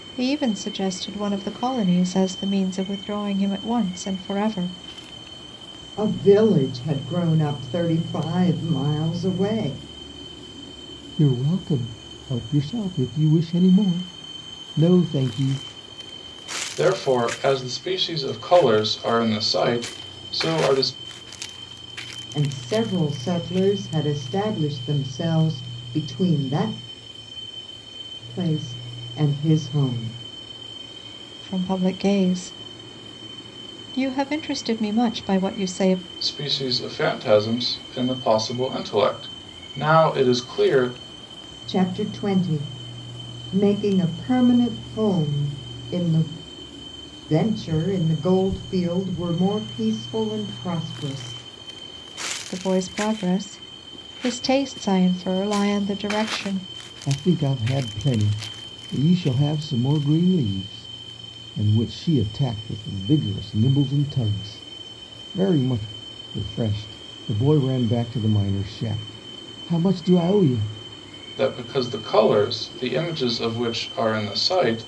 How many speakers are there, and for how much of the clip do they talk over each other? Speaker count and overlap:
four, no overlap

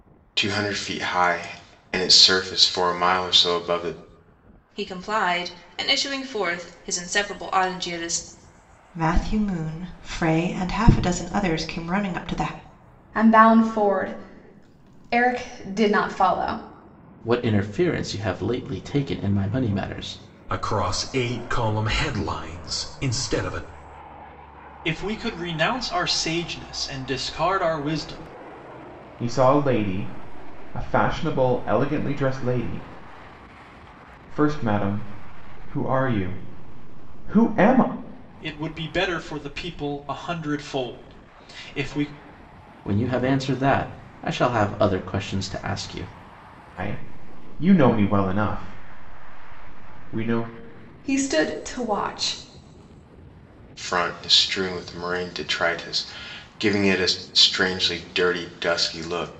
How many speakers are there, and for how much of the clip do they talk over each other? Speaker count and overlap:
eight, no overlap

